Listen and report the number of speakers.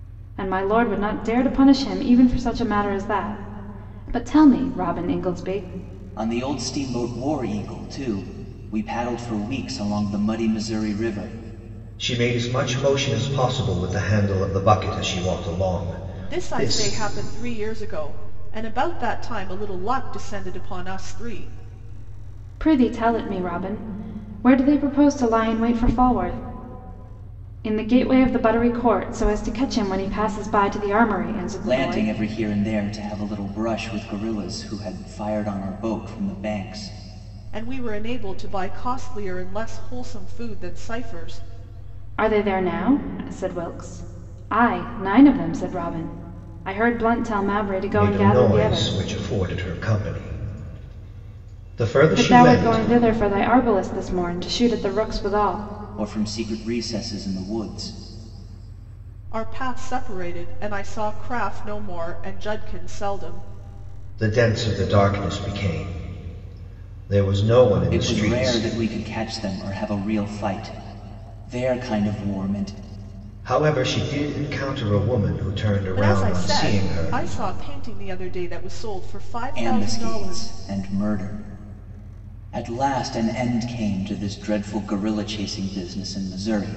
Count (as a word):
four